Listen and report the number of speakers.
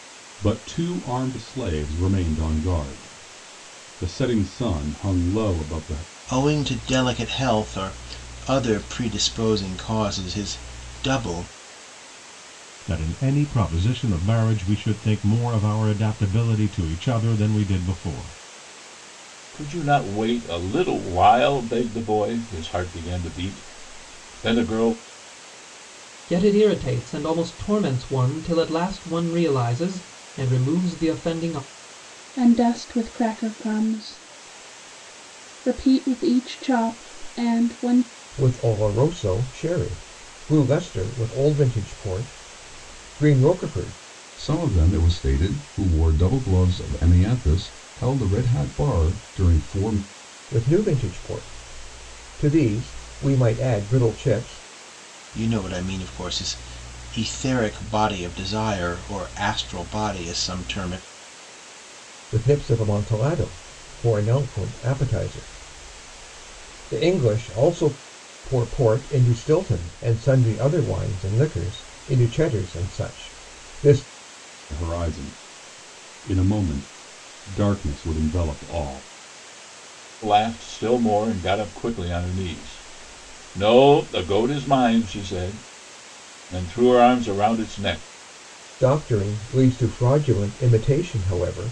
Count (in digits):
8